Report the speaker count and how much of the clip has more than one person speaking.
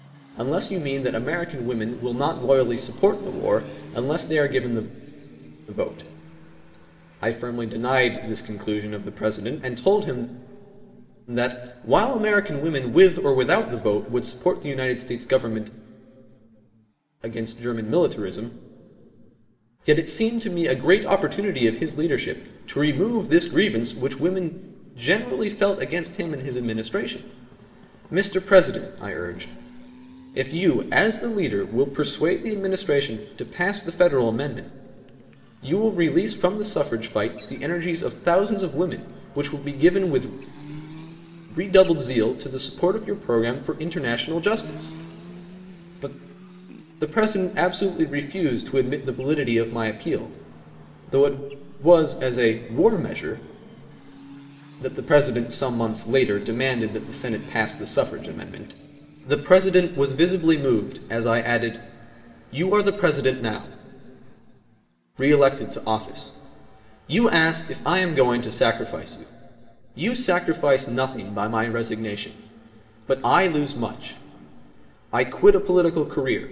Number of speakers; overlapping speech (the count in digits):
1, no overlap